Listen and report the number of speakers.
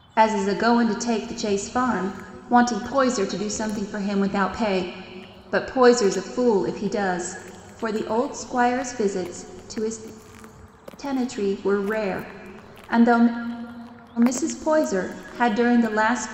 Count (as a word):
one